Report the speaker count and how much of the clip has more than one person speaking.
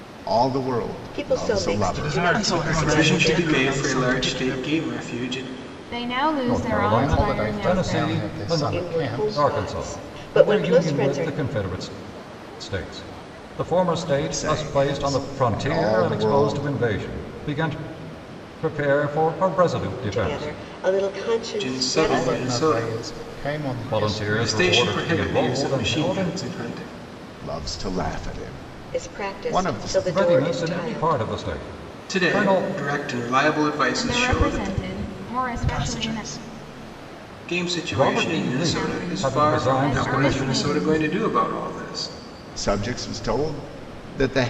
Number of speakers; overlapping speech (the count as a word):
eight, about 52%